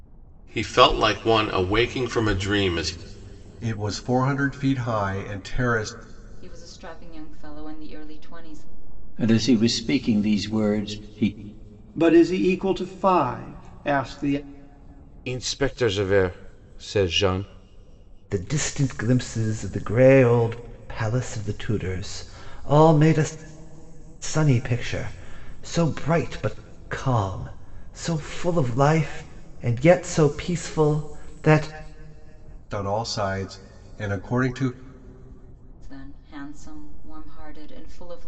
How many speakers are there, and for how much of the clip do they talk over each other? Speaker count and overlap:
7, no overlap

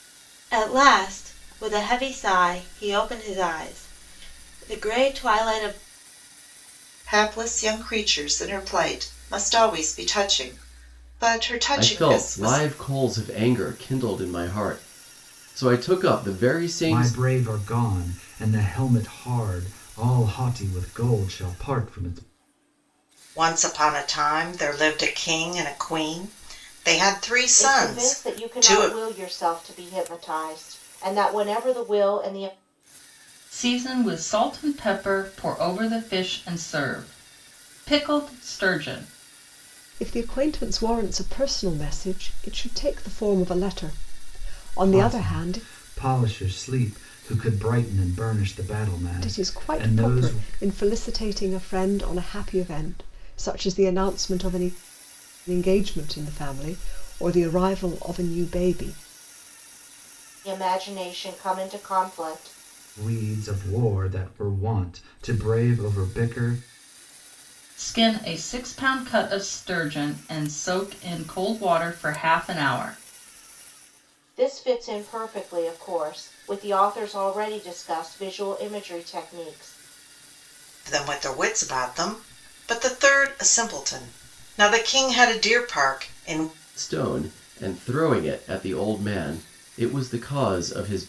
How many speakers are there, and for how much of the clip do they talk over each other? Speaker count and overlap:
8, about 5%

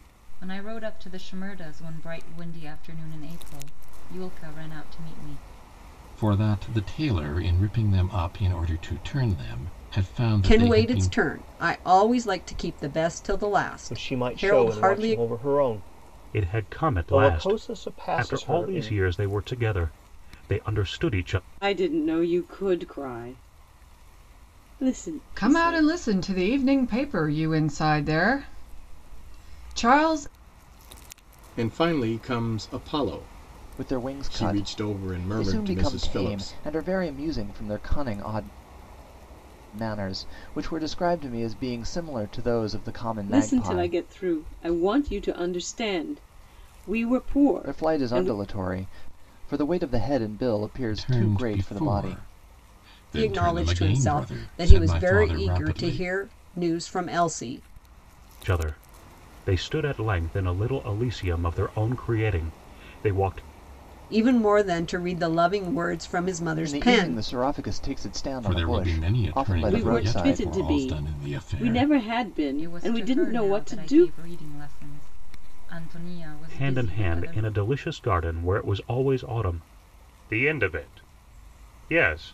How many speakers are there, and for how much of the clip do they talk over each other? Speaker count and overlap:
9, about 25%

